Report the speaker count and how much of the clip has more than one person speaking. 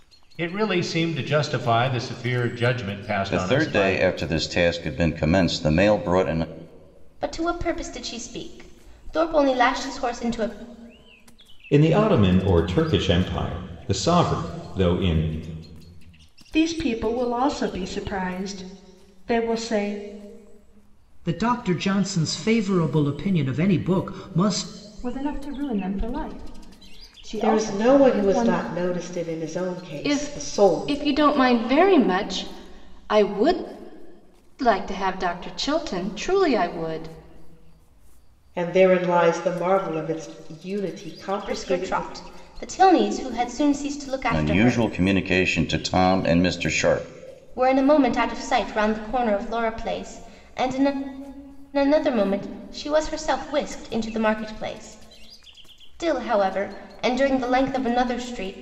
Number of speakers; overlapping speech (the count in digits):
9, about 7%